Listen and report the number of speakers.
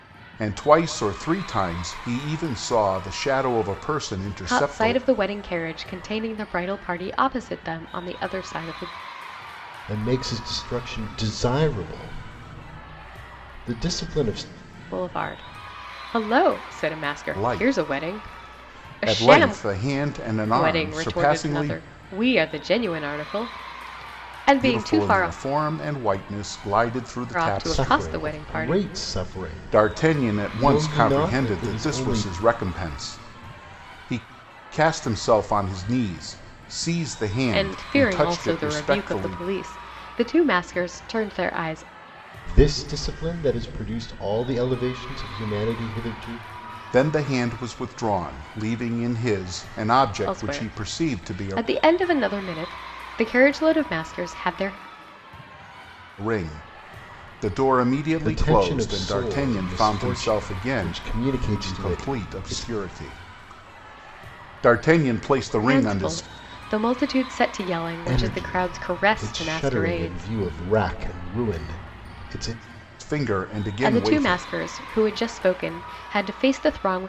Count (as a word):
three